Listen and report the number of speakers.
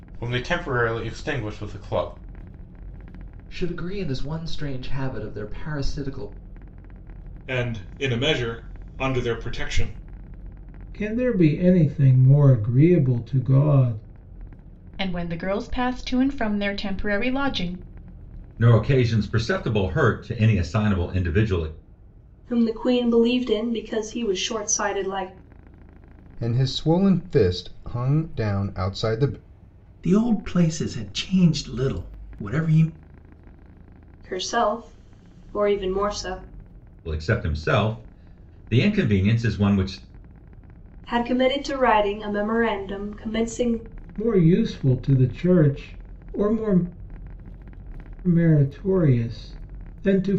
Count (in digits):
9